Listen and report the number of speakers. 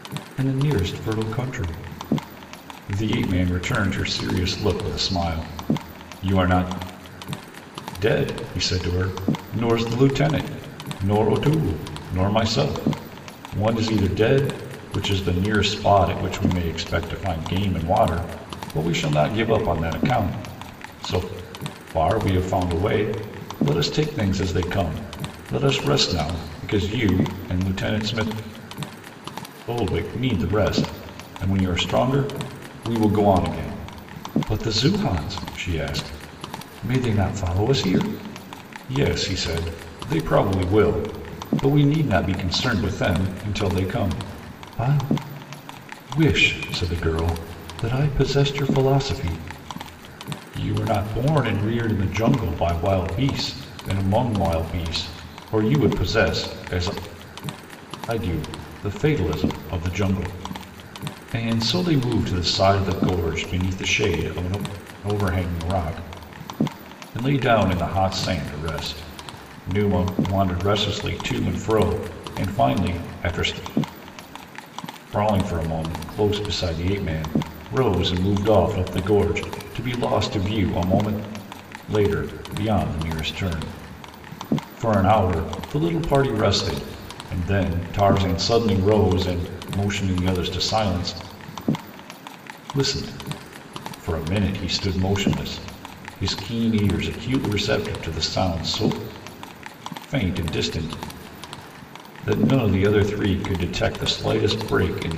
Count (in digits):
1